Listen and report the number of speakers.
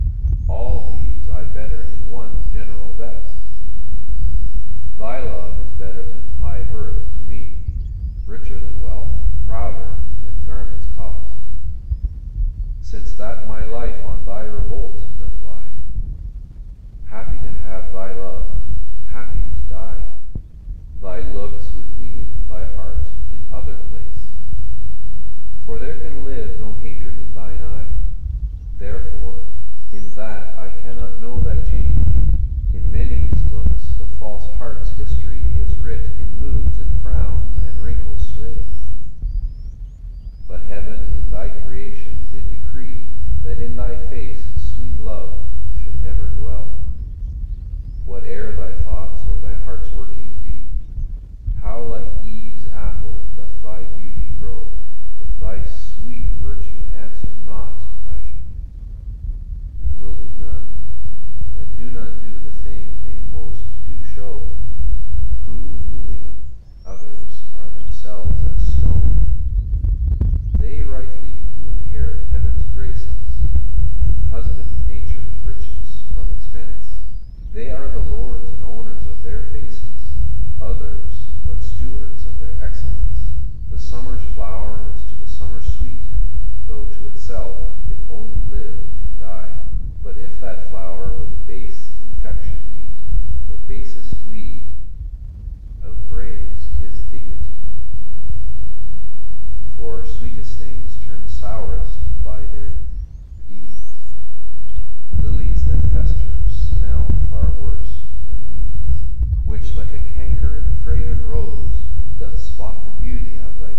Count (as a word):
one